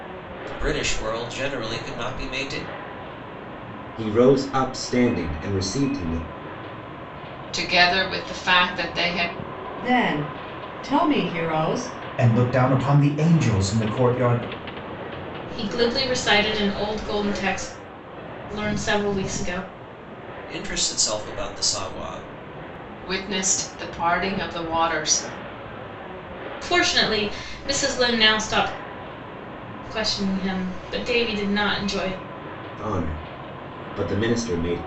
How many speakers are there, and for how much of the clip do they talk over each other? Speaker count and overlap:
six, no overlap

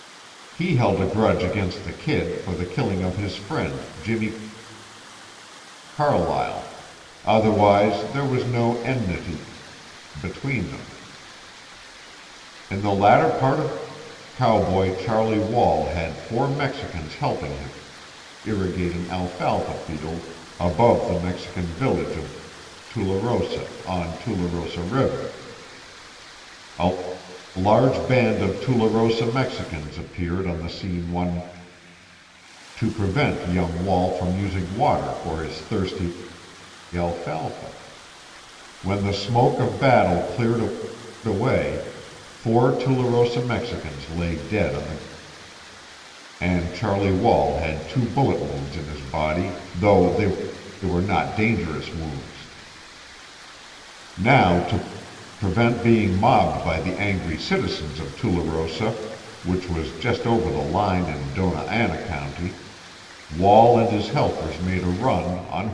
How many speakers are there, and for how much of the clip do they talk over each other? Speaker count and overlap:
one, no overlap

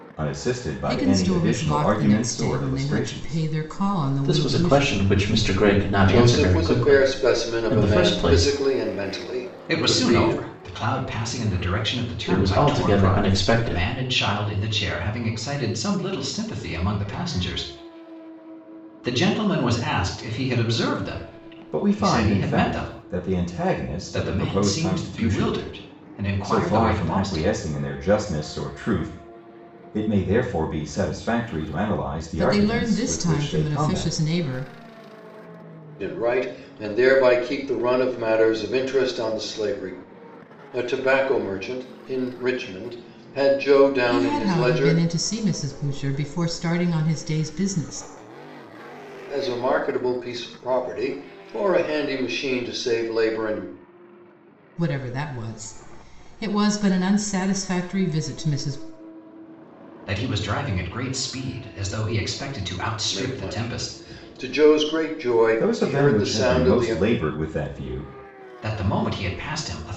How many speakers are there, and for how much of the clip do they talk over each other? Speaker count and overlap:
five, about 27%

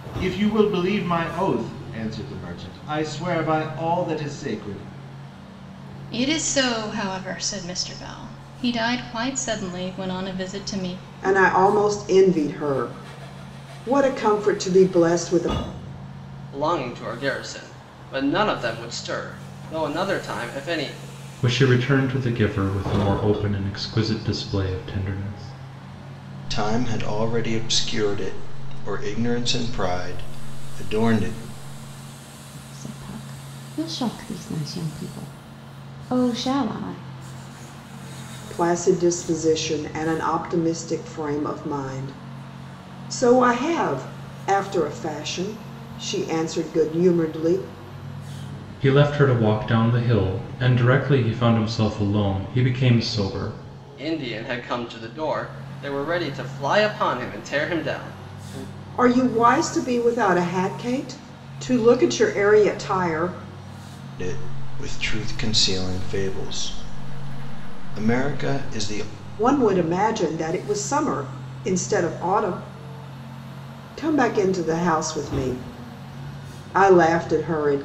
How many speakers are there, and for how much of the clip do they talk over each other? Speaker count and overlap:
seven, no overlap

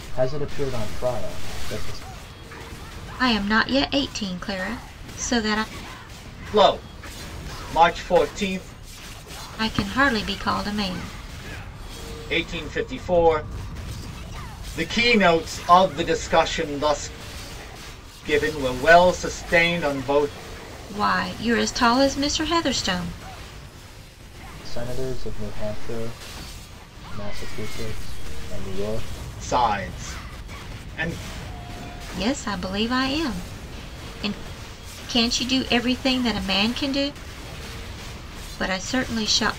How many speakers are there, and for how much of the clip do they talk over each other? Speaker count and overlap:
three, no overlap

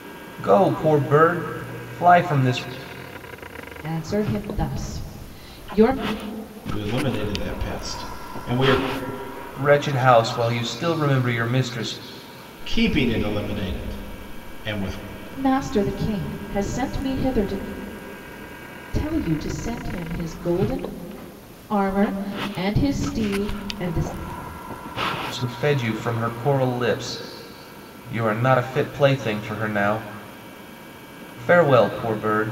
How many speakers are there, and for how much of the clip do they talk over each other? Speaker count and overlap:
three, no overlap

